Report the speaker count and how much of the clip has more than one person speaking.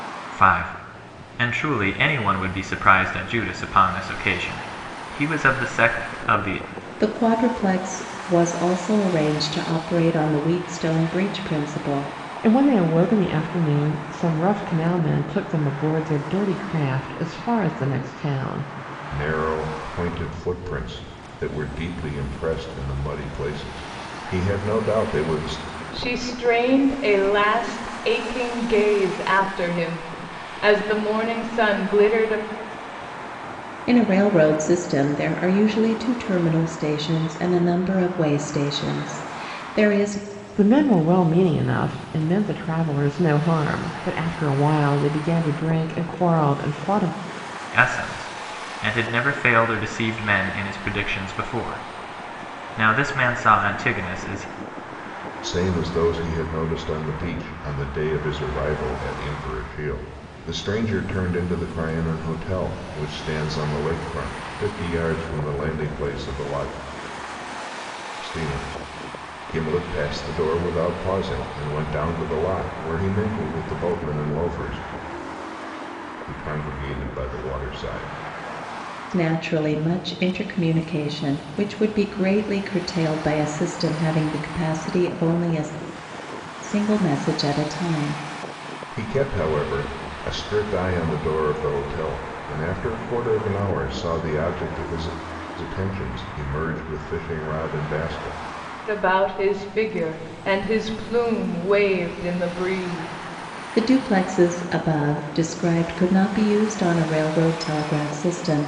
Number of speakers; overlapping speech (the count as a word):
five, no overlap